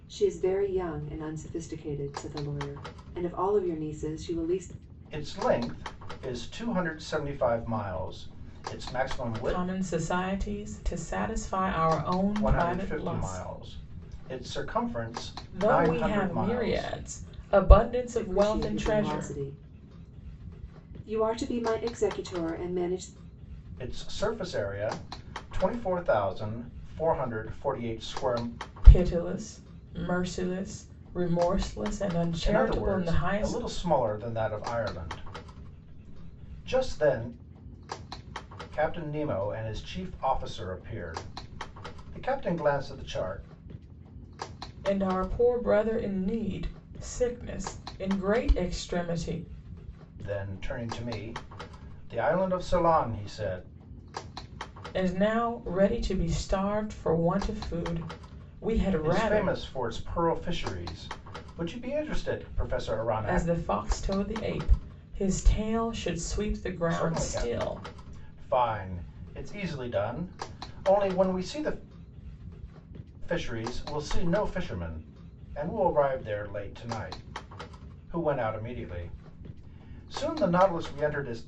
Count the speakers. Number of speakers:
3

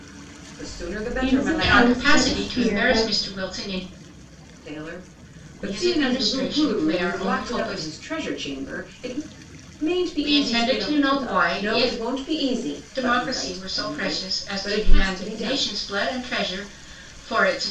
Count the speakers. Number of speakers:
3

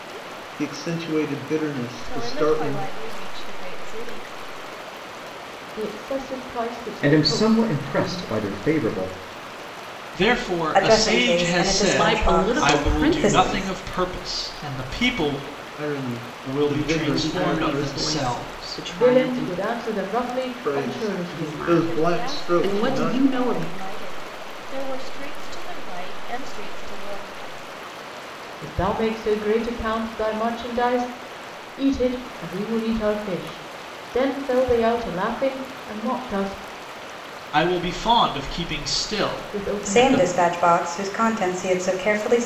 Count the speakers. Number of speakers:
7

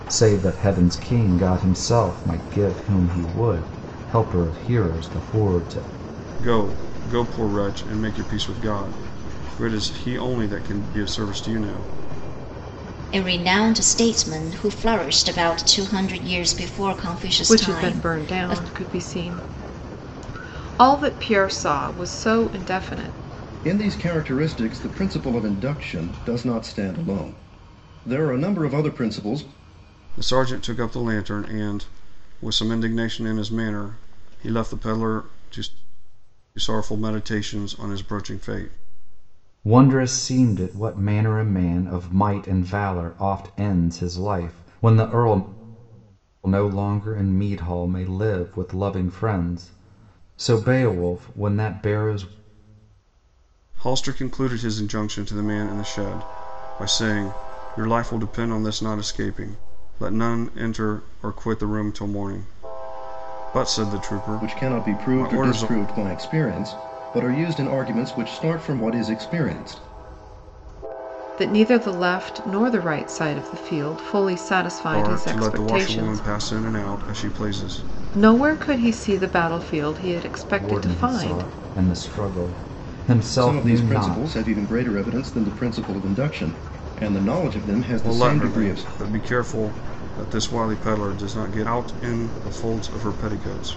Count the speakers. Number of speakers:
5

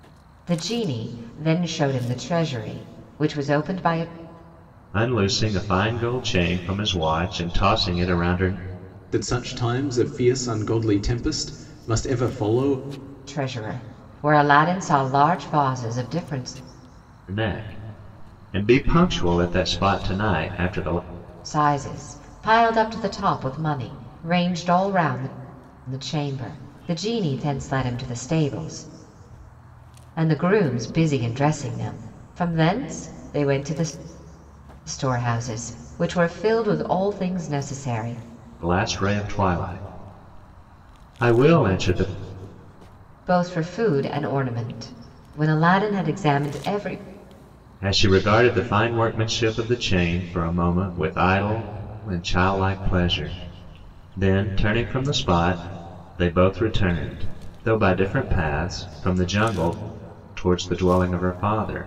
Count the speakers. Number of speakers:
3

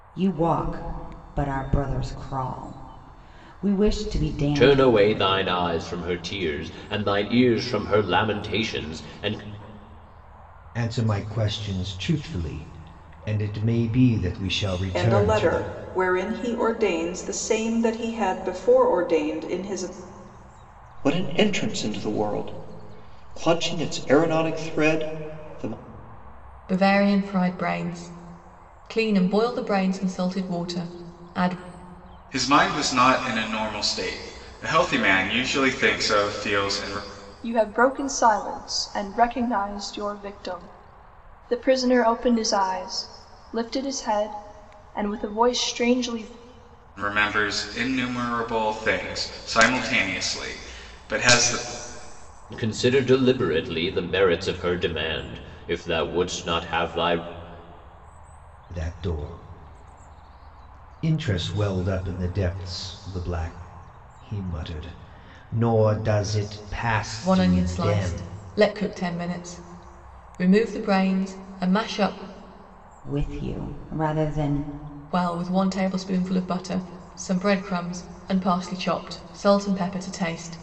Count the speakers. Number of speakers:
8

